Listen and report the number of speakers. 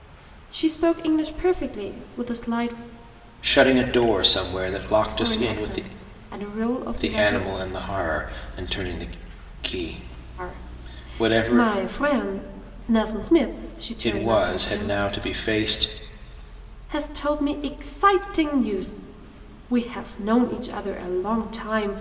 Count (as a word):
two